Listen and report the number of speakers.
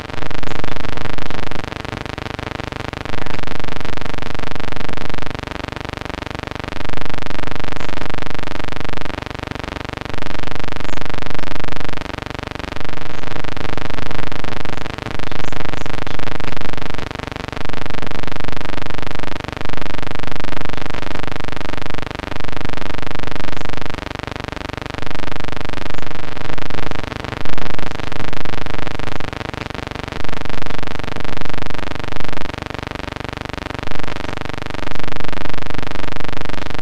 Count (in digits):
1